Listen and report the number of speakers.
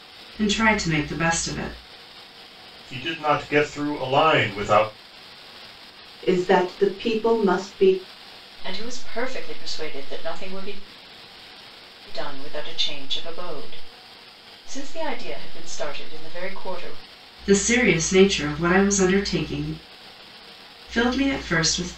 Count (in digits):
4